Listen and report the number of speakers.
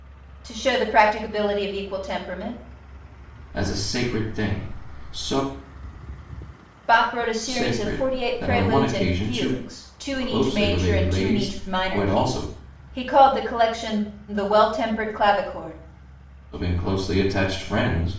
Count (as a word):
two